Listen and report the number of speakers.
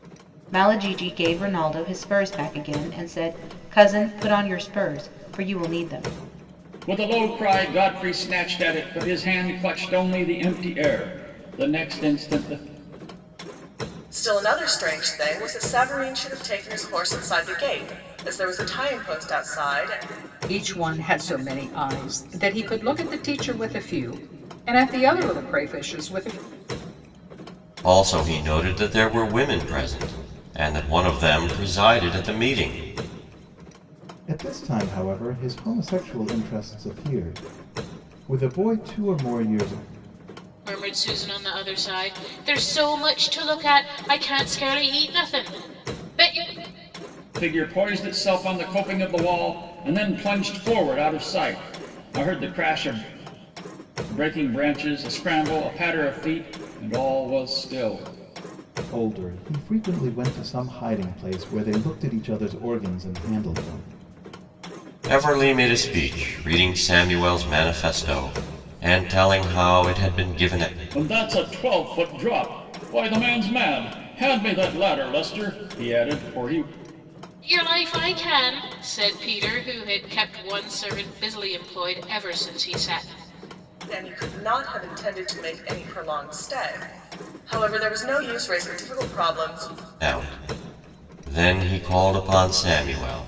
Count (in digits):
7